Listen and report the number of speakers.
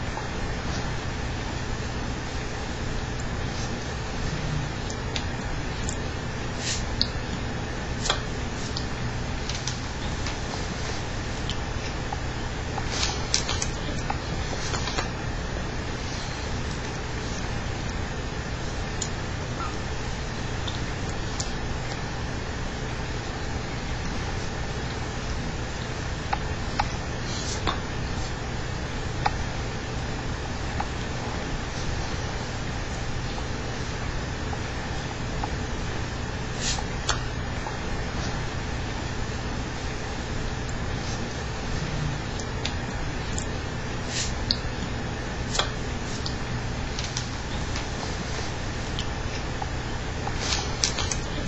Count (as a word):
zero